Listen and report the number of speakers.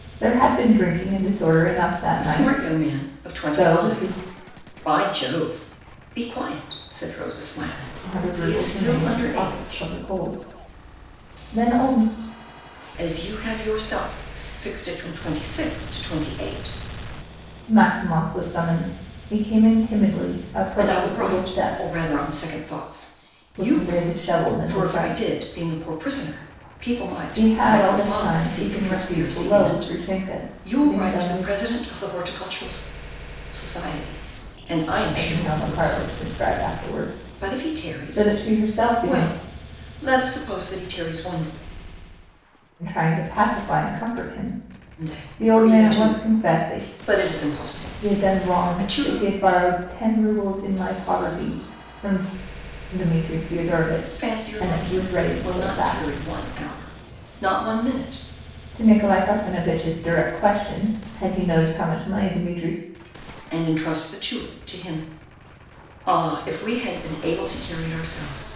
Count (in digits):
2